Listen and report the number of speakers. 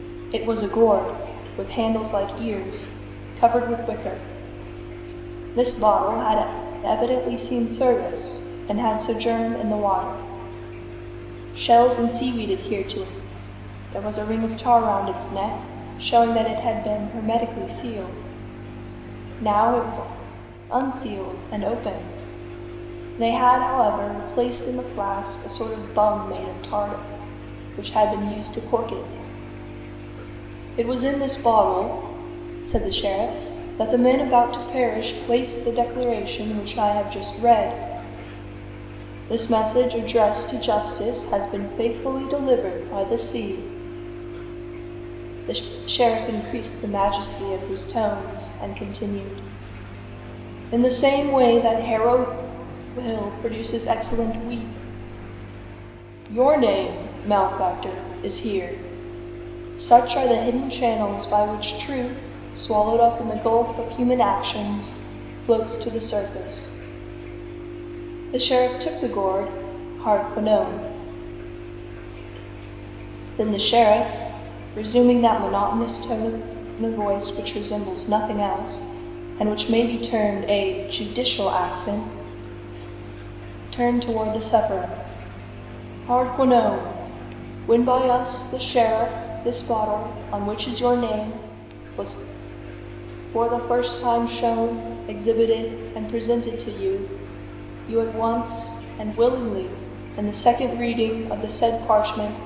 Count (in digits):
1